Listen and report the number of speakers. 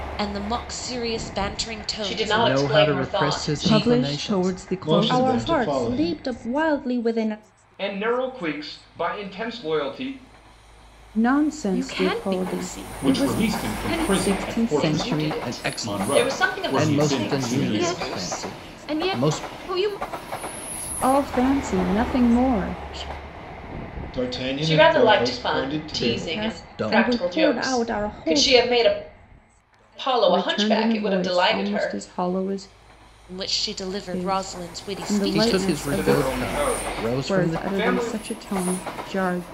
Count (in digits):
10